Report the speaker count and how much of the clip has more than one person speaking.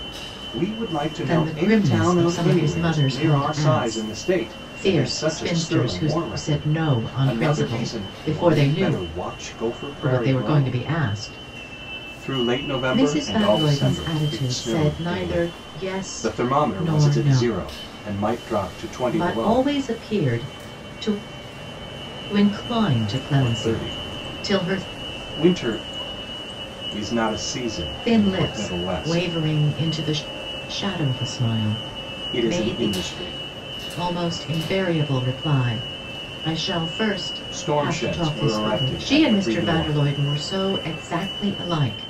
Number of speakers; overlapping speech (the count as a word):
two, about 45%